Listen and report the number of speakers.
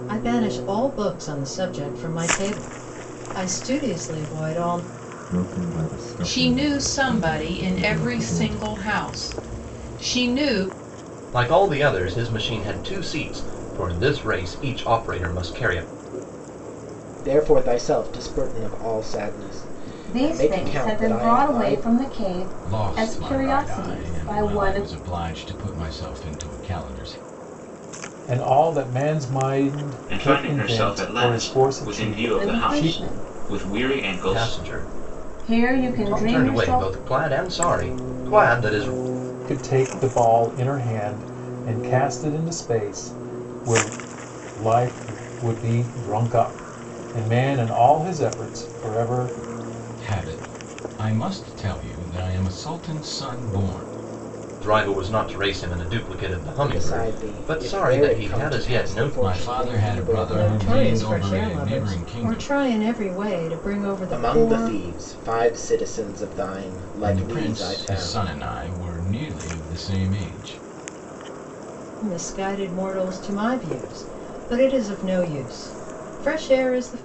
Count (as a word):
nine